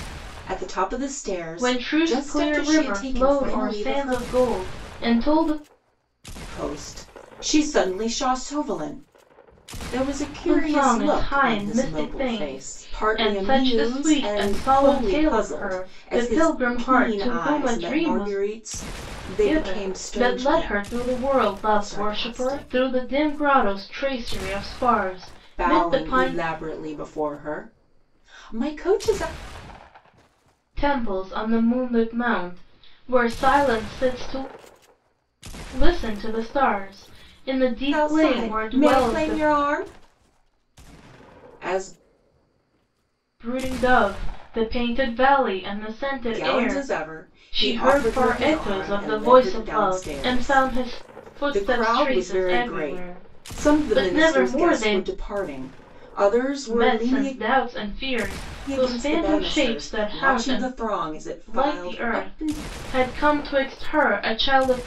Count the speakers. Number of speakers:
2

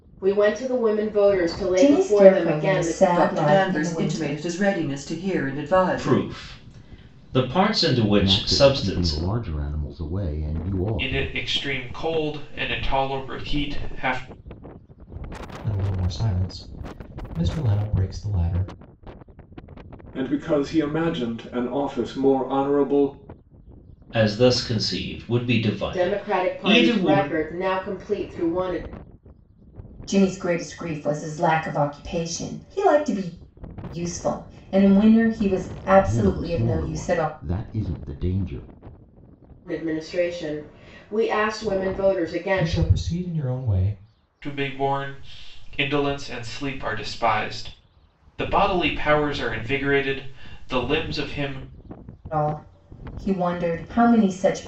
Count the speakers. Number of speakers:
8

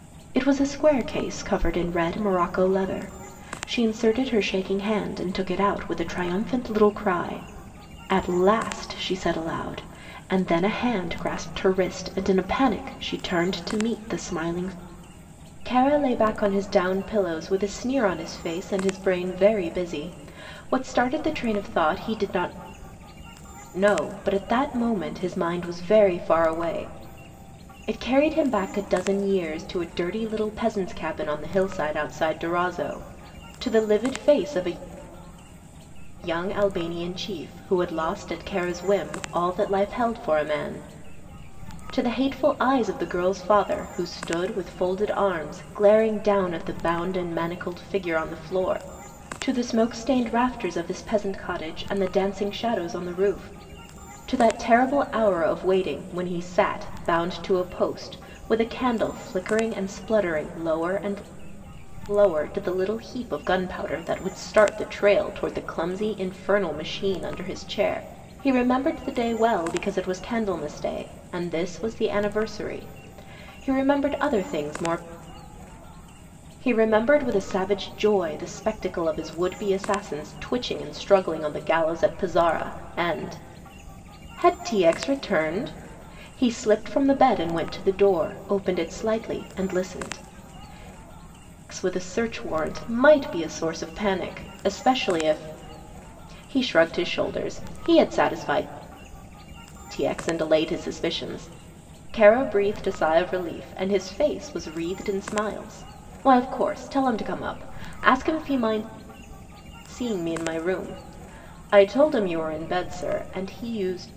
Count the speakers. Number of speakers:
1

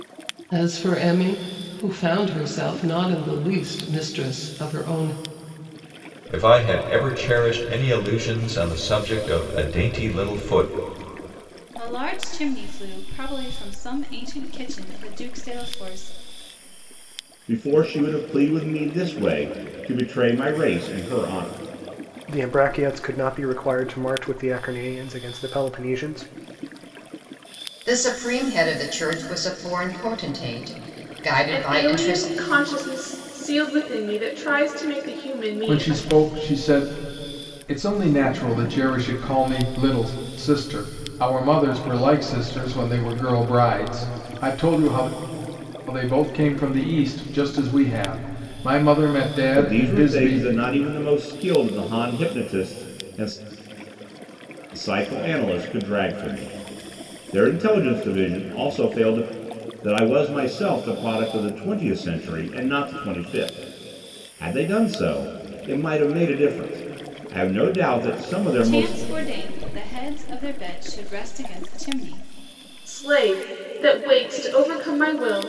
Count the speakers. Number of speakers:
8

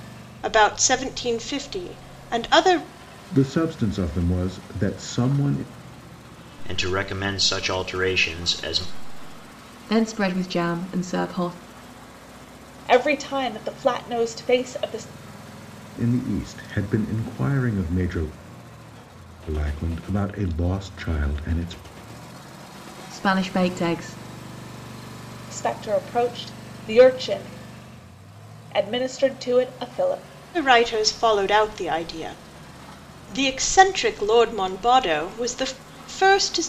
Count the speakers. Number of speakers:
5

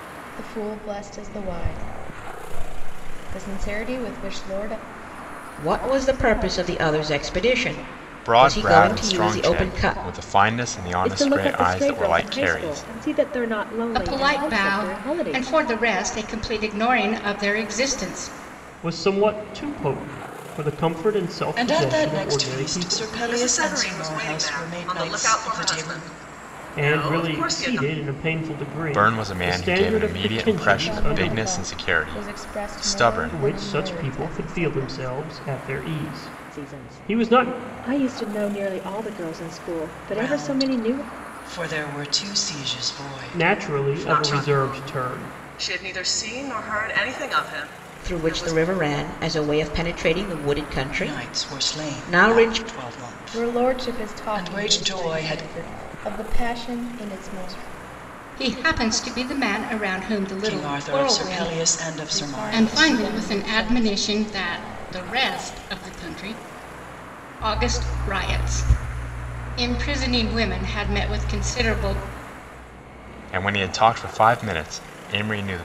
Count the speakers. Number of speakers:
8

